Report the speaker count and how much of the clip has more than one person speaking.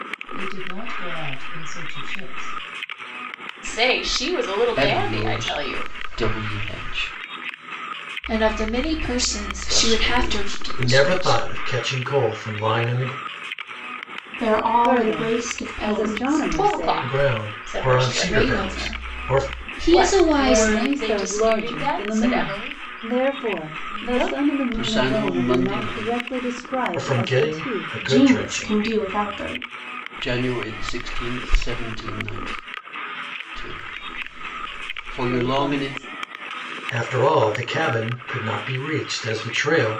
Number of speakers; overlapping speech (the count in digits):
8, about 39%